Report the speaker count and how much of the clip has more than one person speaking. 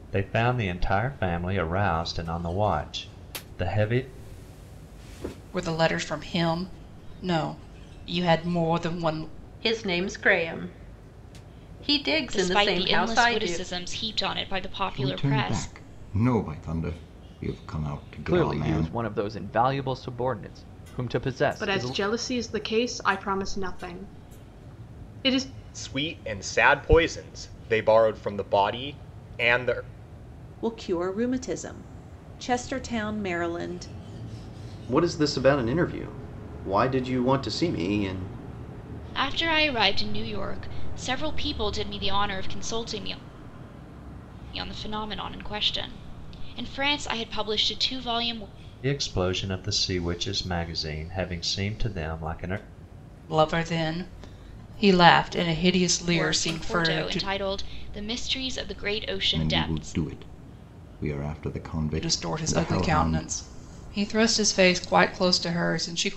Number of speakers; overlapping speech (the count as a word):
ten, about 10%